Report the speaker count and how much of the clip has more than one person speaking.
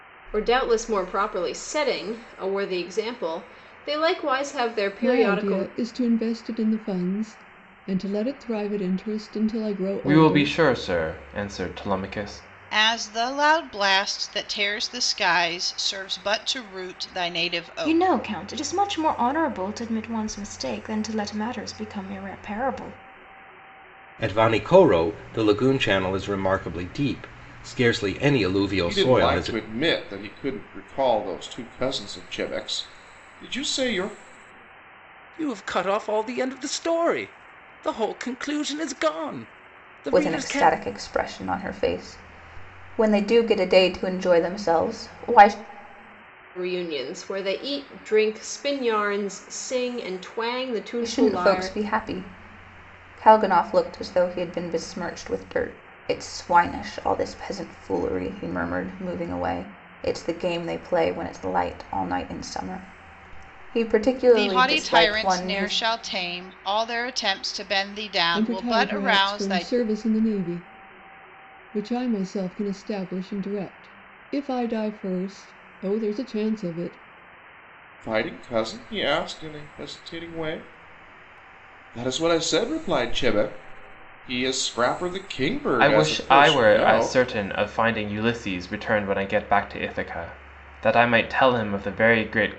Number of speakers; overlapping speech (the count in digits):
9, about 9%